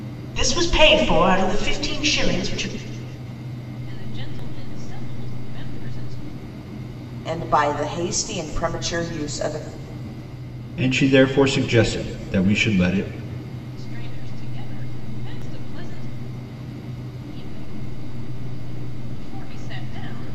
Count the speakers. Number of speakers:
four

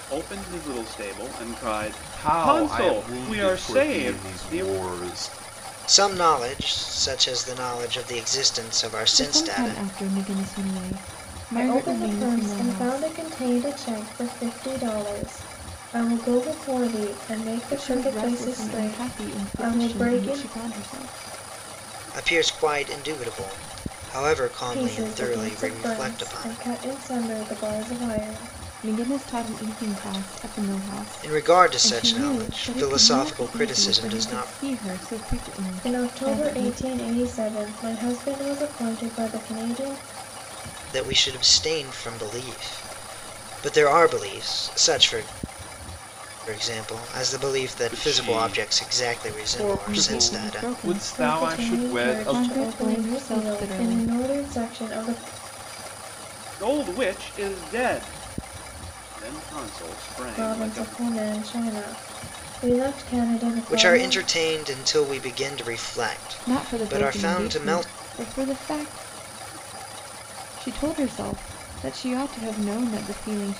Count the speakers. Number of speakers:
five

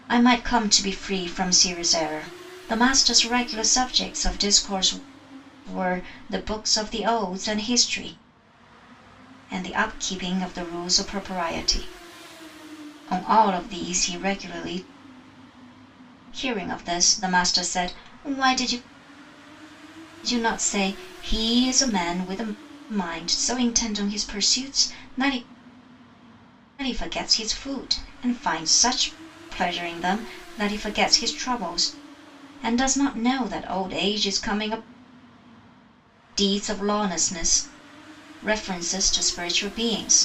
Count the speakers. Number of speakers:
one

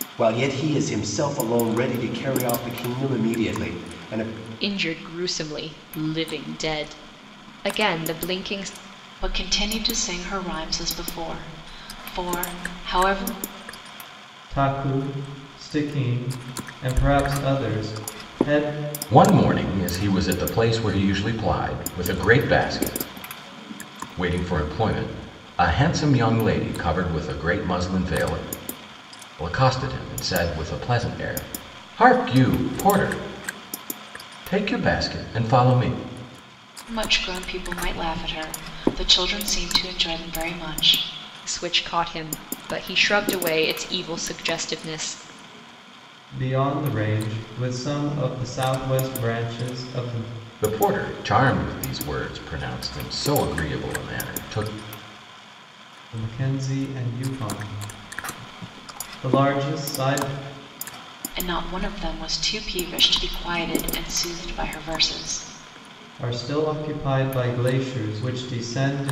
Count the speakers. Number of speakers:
five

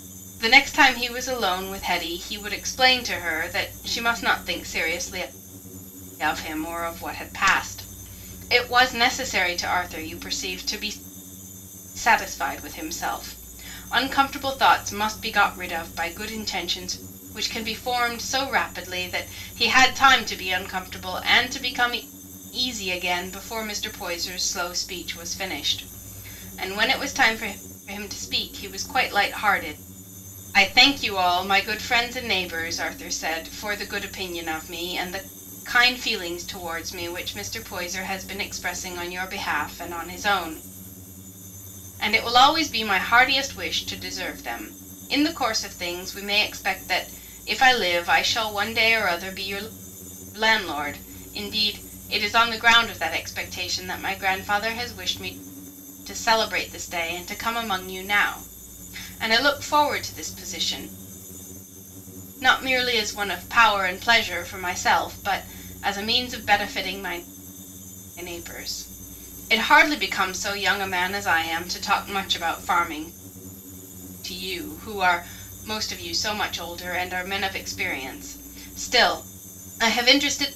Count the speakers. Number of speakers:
one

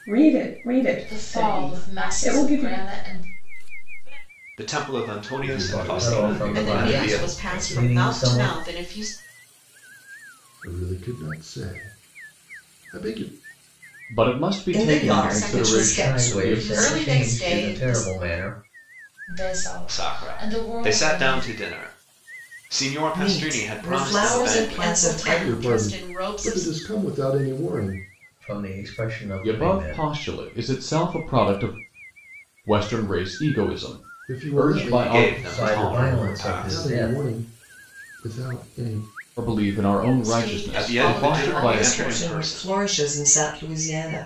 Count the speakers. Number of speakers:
ten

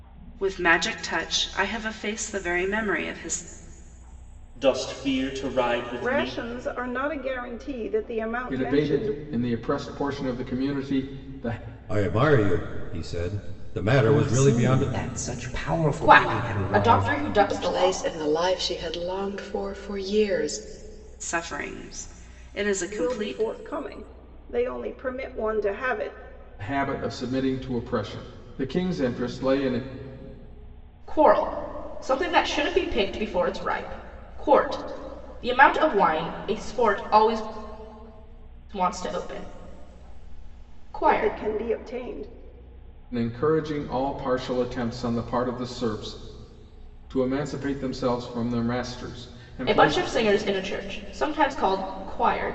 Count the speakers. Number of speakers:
eight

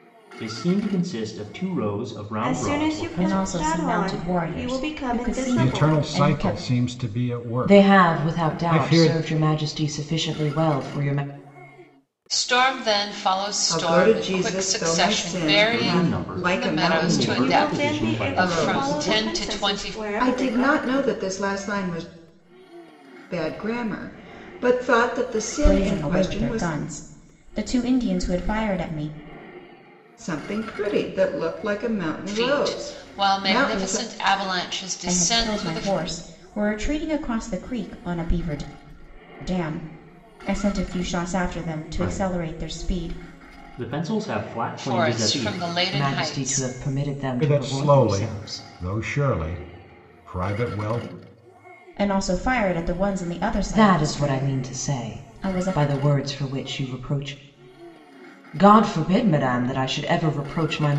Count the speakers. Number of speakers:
seven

